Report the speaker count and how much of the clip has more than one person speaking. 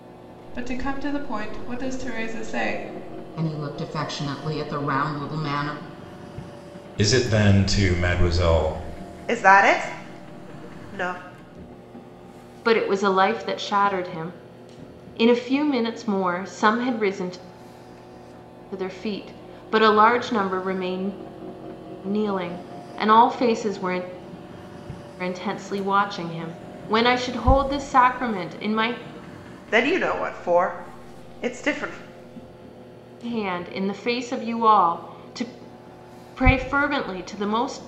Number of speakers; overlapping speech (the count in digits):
5, no overlap